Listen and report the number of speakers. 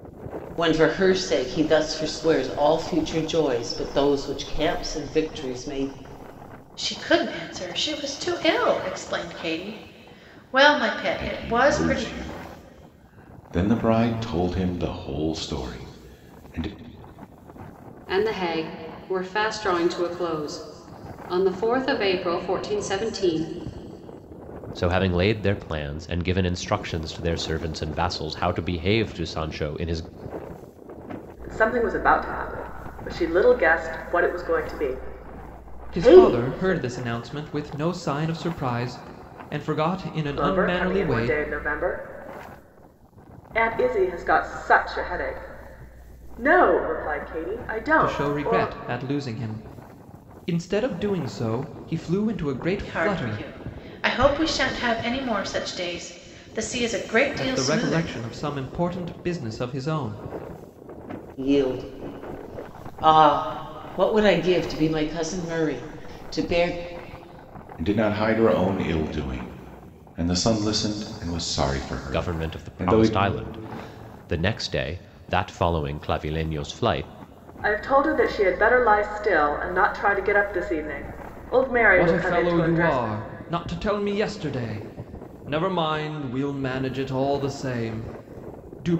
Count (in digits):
7